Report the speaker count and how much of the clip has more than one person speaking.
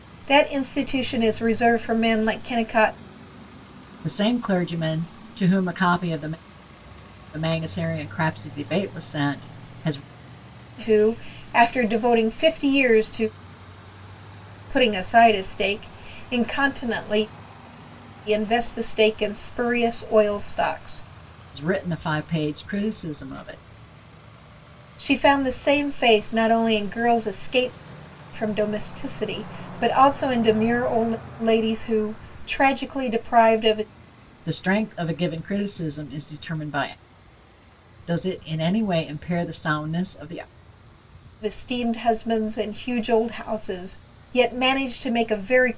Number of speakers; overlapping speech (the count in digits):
2, no overlap